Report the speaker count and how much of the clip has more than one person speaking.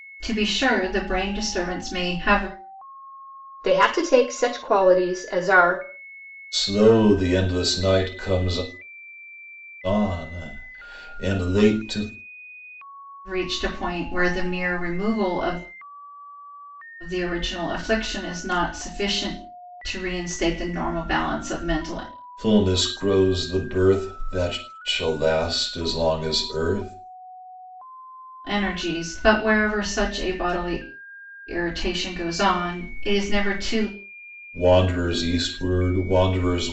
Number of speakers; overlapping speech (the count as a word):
three, no overlap